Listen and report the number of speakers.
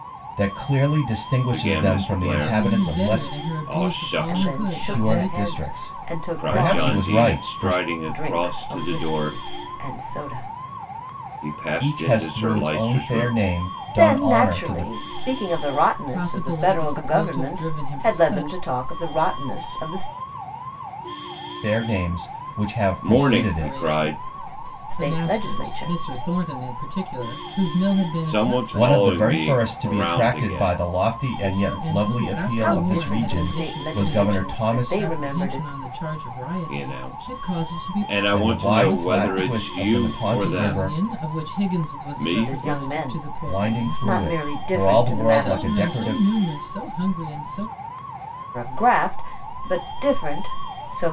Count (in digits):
4